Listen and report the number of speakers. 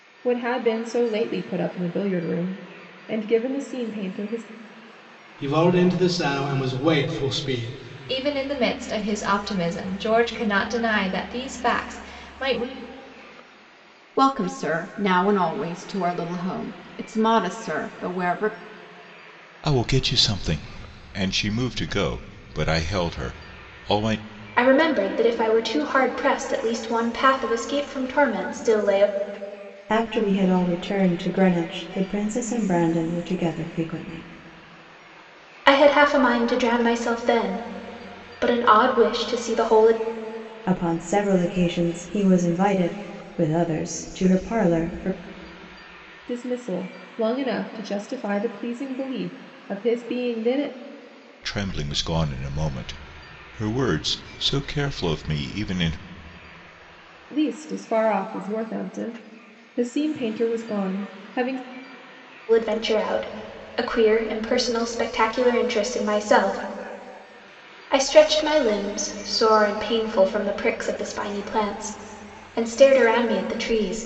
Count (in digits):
7